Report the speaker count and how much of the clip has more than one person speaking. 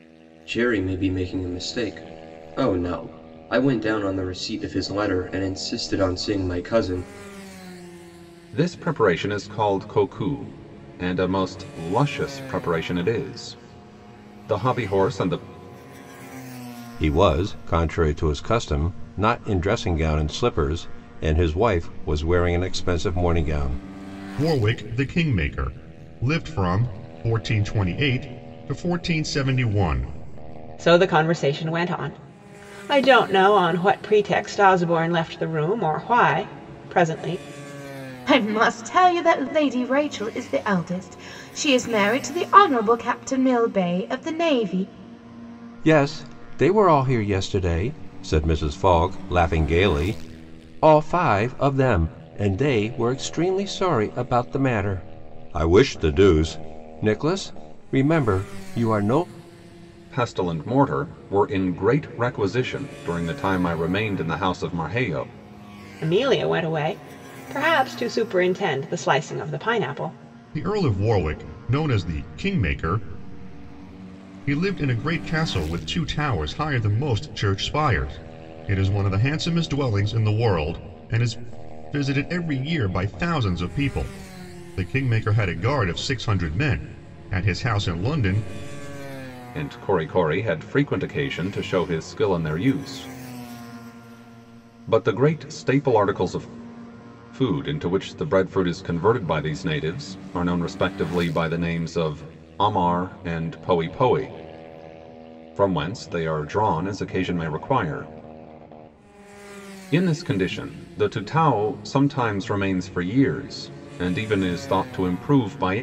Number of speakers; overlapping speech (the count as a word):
six, no overlap